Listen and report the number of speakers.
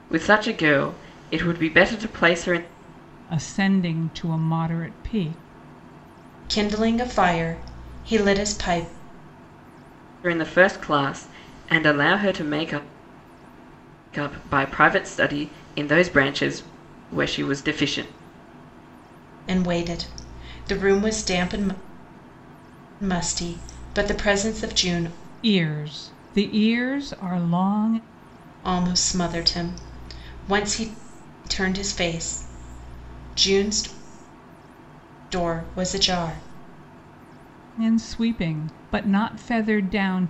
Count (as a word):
three